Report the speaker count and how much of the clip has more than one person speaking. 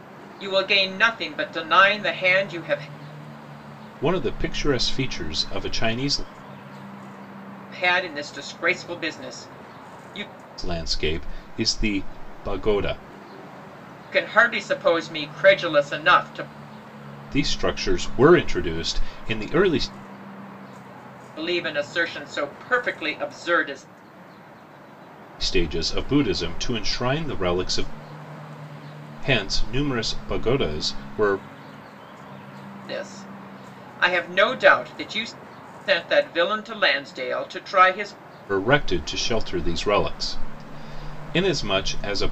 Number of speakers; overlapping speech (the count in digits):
2, no overlap